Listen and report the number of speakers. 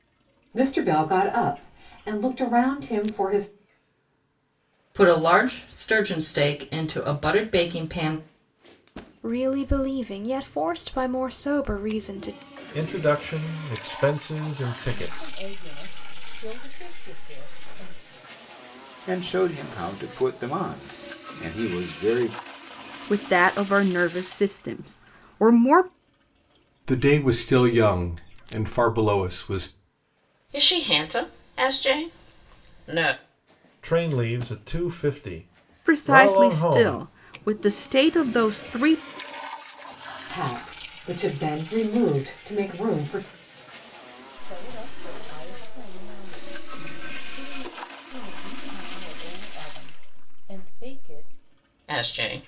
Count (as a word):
nine